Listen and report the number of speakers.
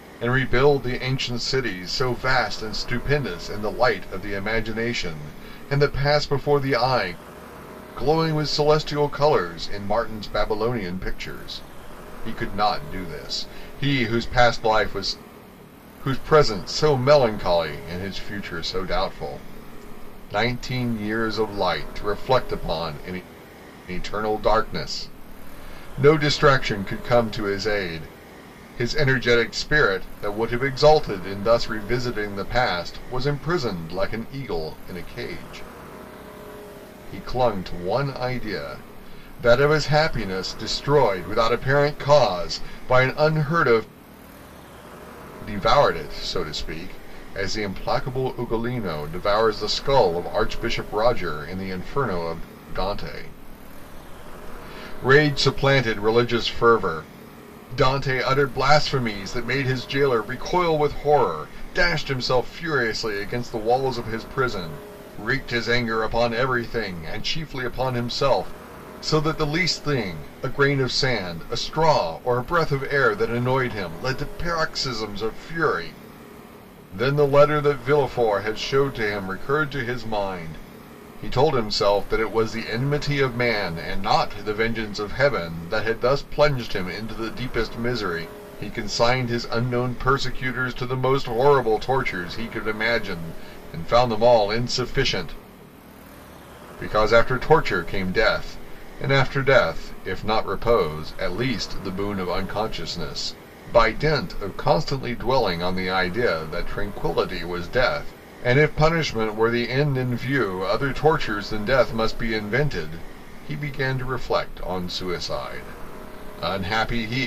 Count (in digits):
1